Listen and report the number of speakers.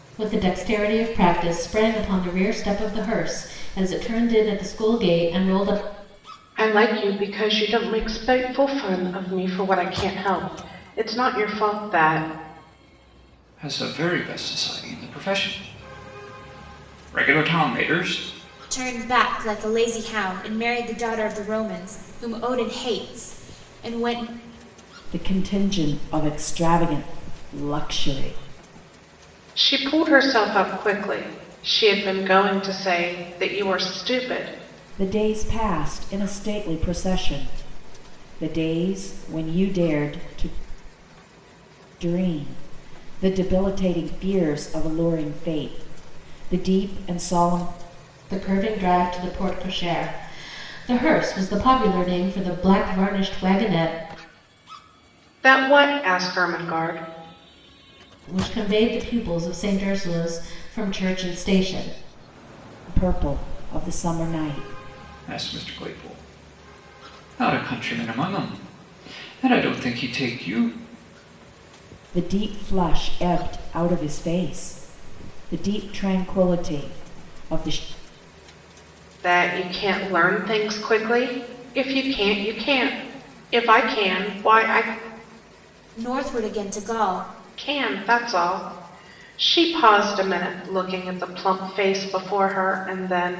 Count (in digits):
5